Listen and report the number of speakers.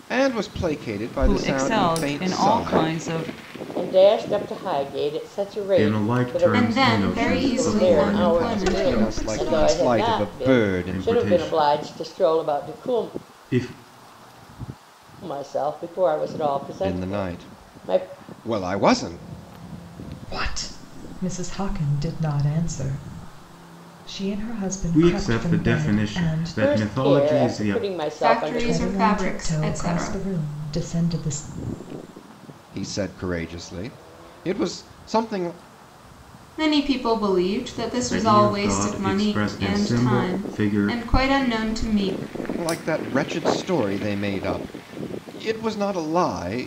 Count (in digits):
6